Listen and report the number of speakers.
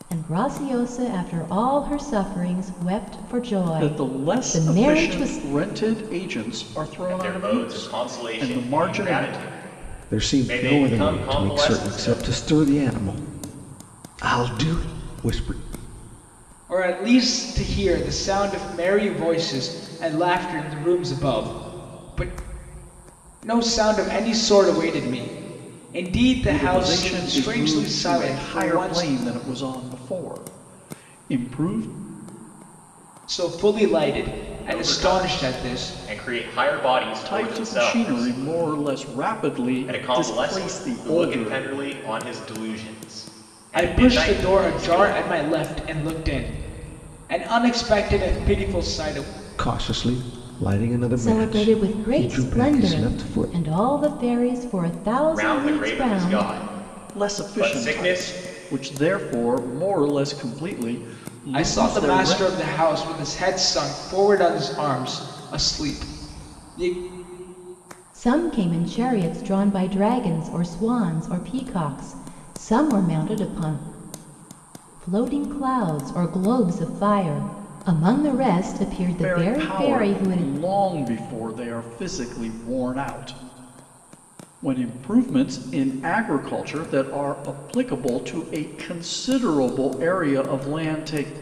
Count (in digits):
5